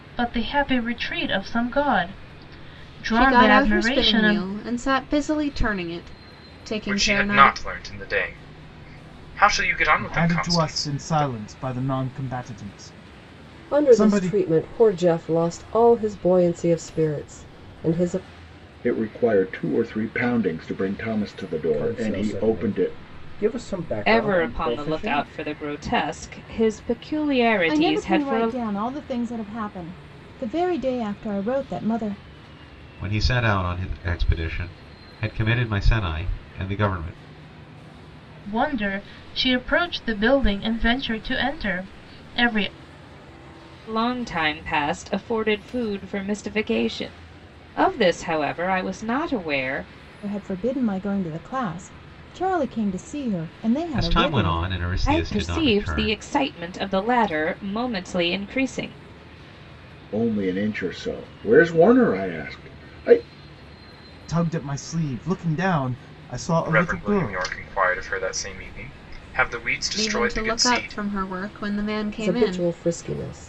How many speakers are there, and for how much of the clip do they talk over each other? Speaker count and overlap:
10, about 16%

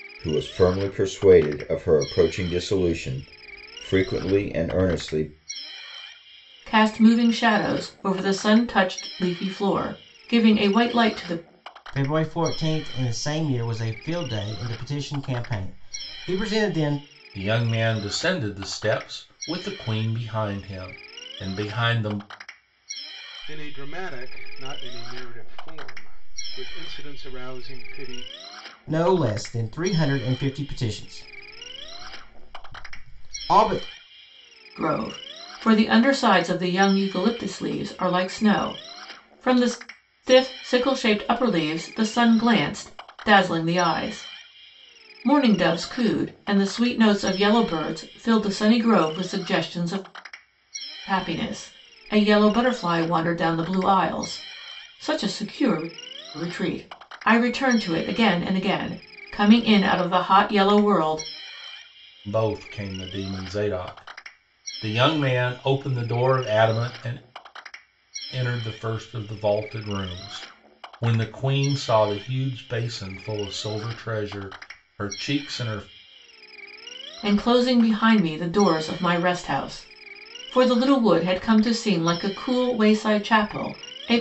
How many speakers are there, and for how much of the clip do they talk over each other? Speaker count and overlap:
5, no overlap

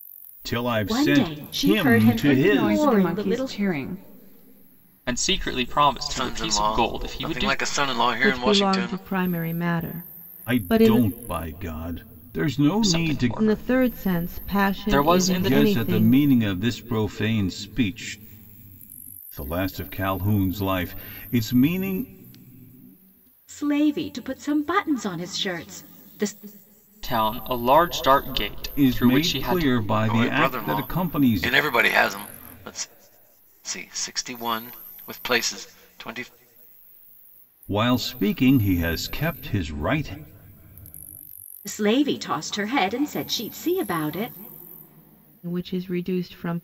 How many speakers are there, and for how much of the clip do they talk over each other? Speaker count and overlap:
6, about 24%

